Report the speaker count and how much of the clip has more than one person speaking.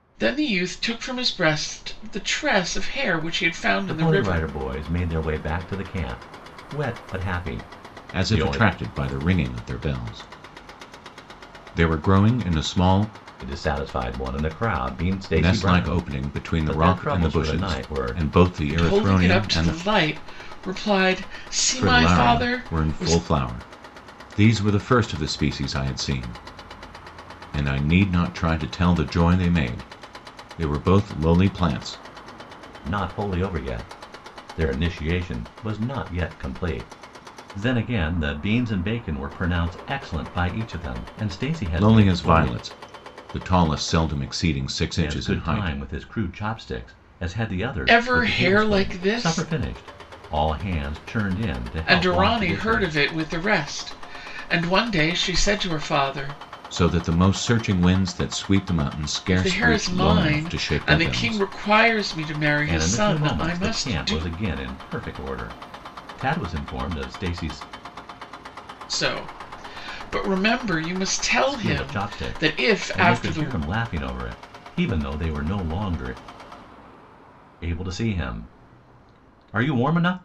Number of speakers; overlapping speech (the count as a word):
three, about 21%